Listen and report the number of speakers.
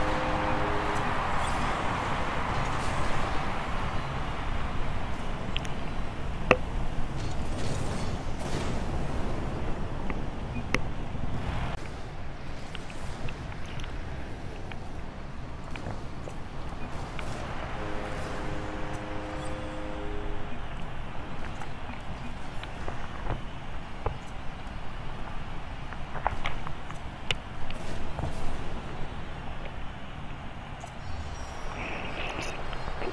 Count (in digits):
0